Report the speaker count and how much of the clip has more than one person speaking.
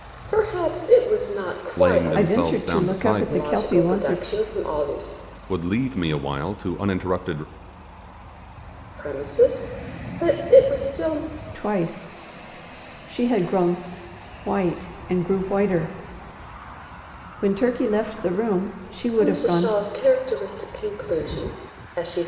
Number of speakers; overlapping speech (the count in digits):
3, about 14%